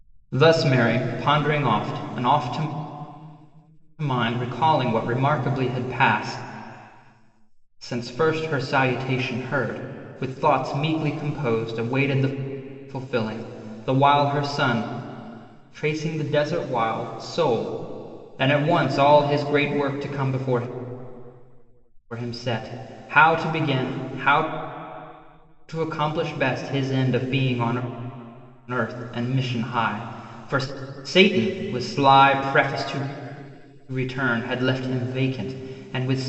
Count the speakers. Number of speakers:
1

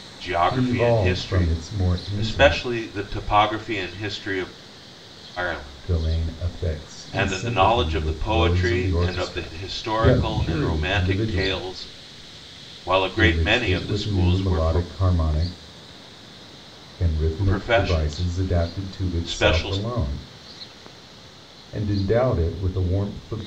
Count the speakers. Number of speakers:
2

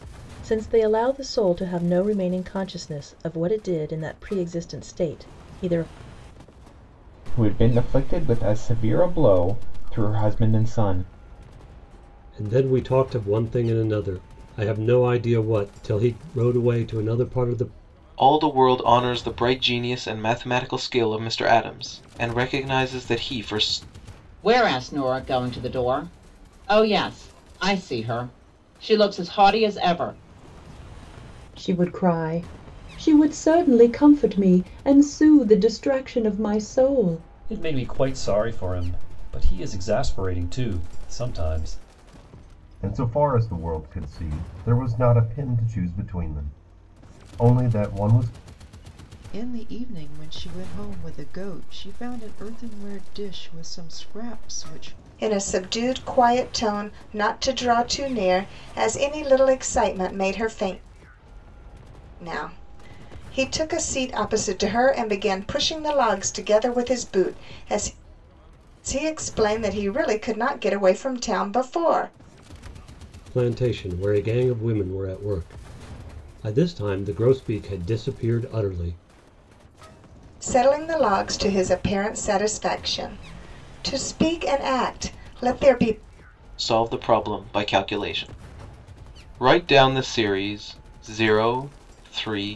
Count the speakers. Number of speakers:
10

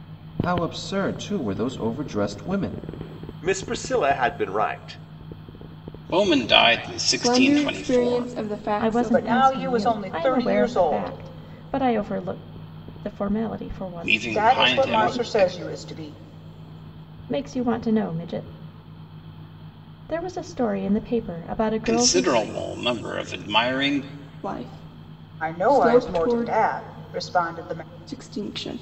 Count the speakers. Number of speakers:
6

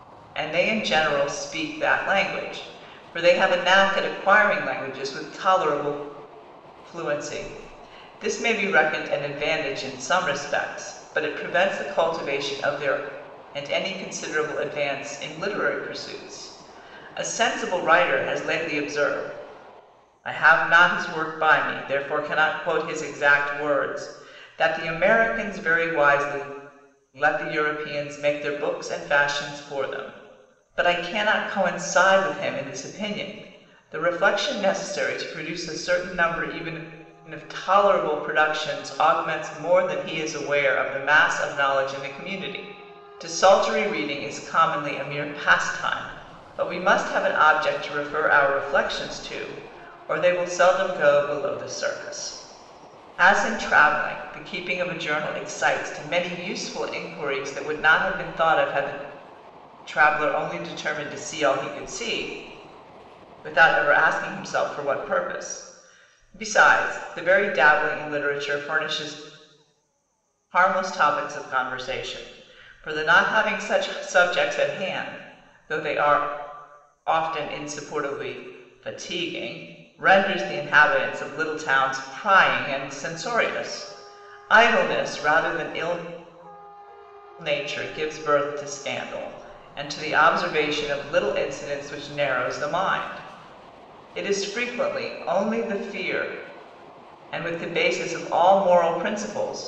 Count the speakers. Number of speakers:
1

